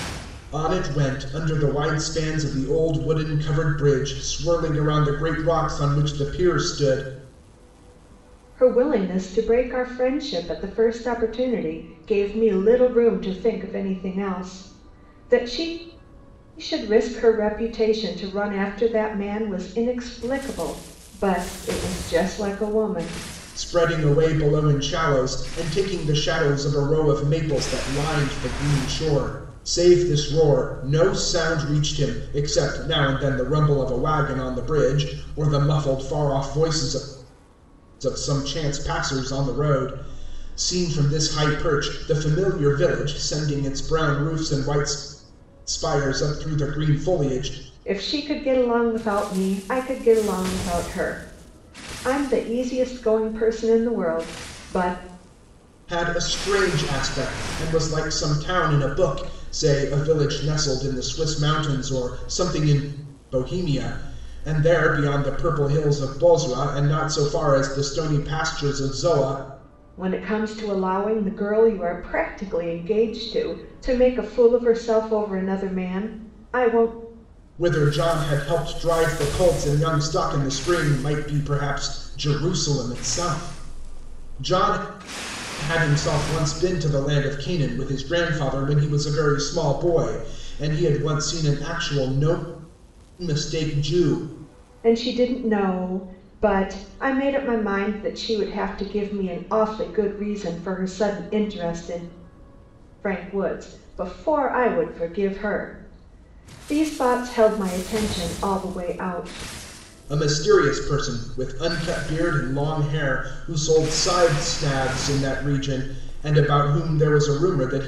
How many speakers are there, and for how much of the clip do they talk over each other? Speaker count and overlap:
2, no overlap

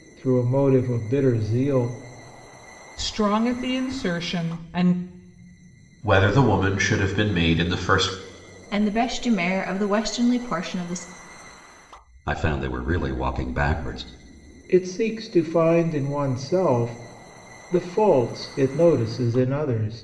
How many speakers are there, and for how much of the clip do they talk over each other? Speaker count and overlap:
5, no overlap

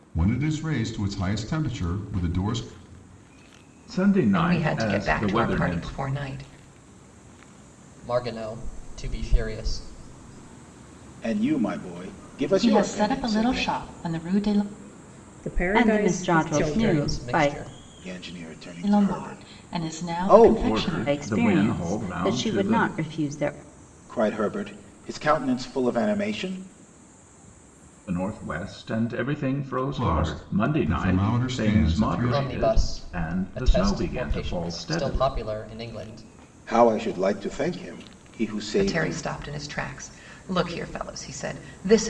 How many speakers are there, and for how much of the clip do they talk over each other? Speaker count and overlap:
8, about 34%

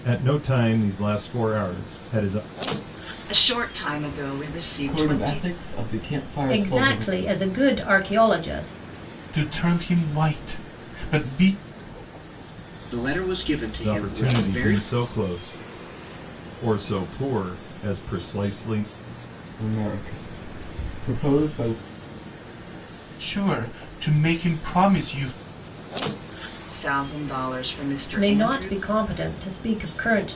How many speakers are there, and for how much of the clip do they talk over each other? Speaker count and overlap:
6, about 10%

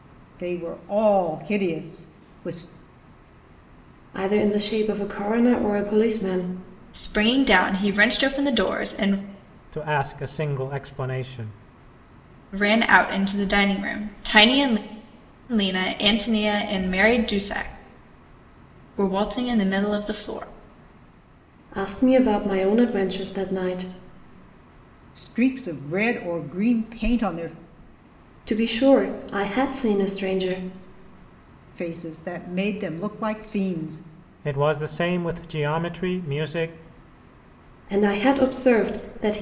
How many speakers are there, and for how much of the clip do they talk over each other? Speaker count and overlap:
4, no overlap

